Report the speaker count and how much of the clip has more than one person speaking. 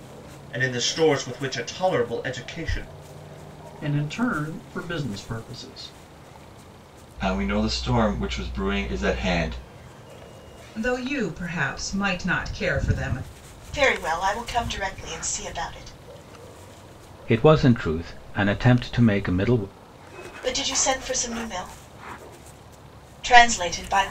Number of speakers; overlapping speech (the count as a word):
six, no overlap